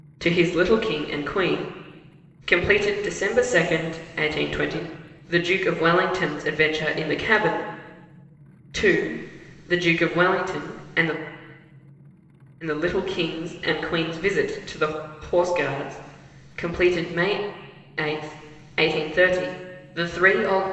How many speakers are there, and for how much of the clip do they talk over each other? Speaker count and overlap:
1, no overlap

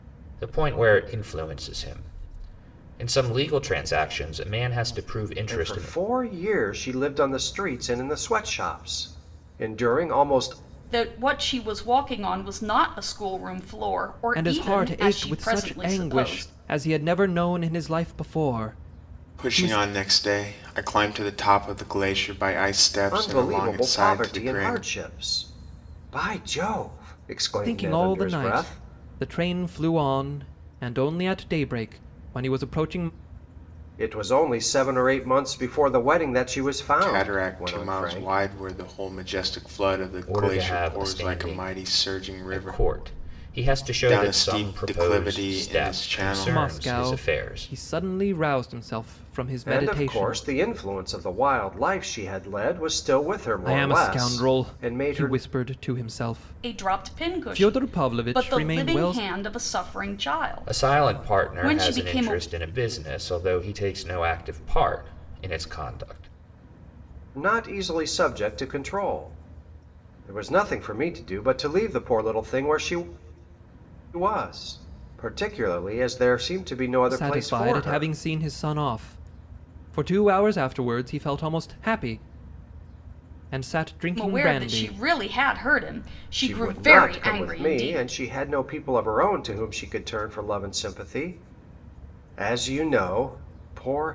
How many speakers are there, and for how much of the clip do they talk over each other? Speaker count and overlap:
5, about 26%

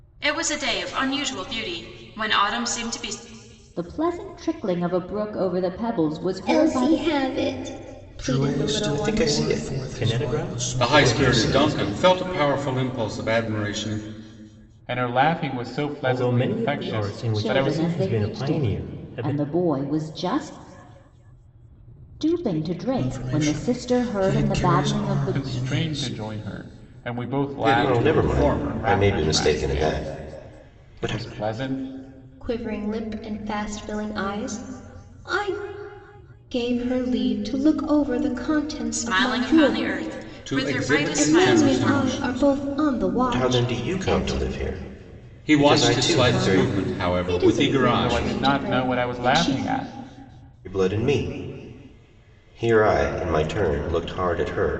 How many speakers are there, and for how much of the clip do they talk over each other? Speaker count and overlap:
8, about 42%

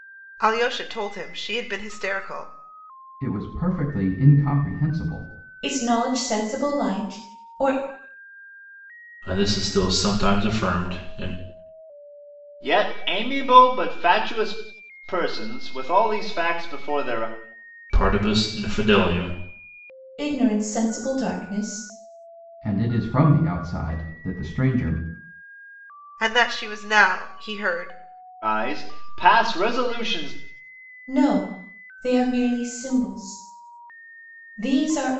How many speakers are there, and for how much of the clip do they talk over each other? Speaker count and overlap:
5, no overlap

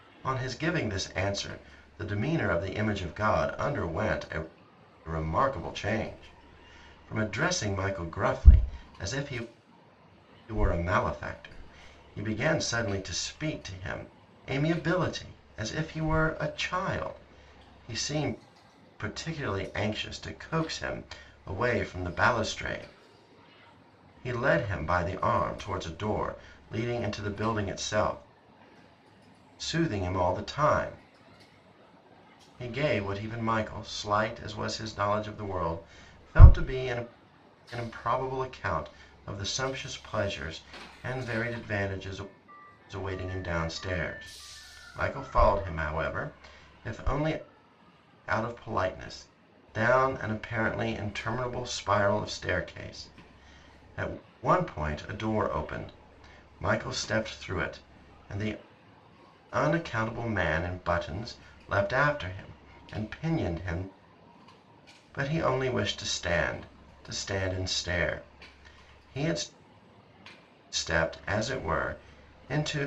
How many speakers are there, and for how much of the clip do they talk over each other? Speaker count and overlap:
1, no overlap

